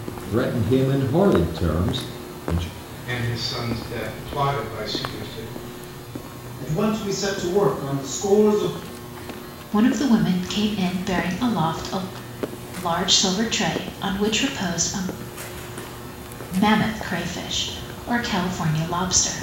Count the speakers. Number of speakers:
four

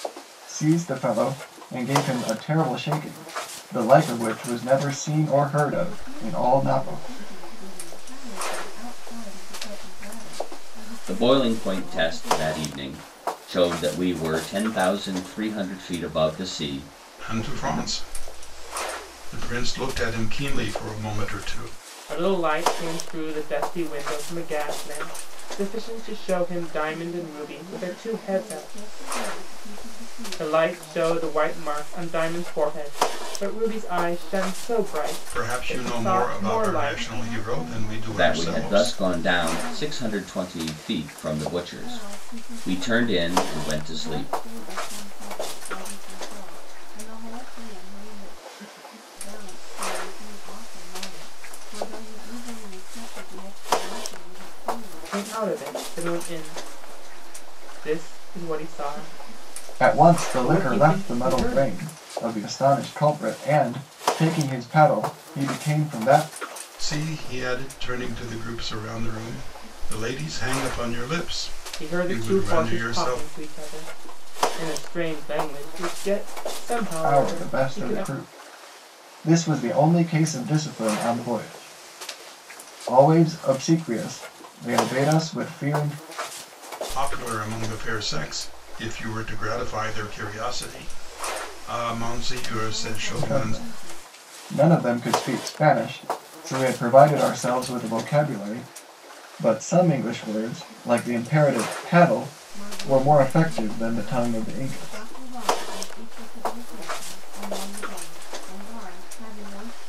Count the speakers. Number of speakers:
five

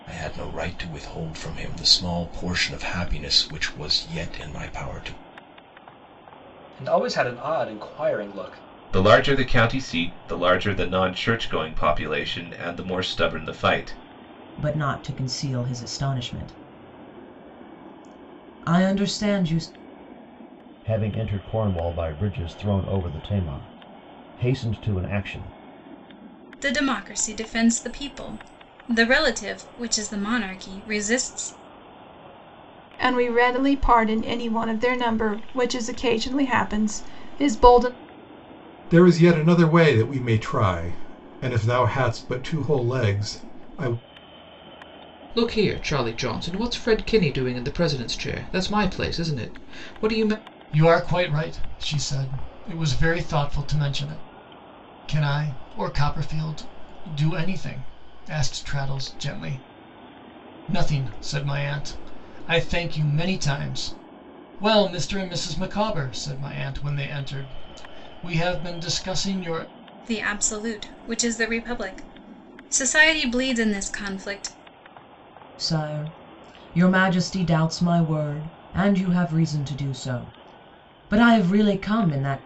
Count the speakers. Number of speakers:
ten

